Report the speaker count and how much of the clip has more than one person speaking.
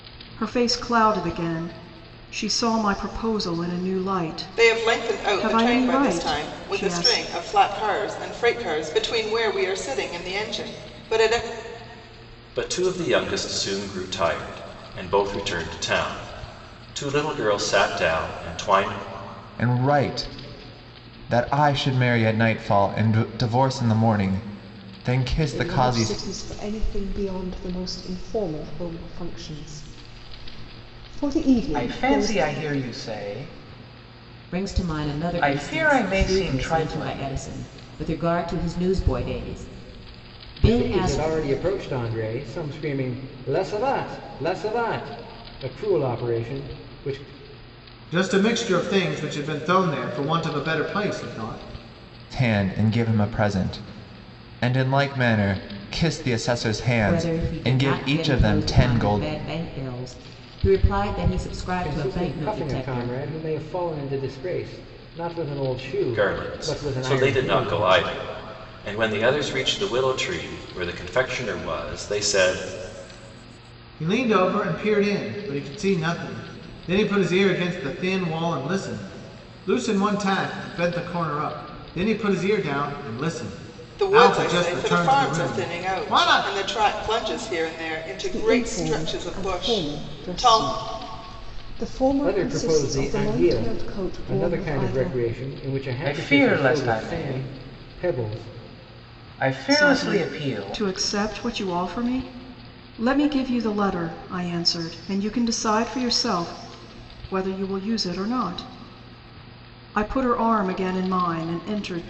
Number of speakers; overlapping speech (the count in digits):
9, about 22%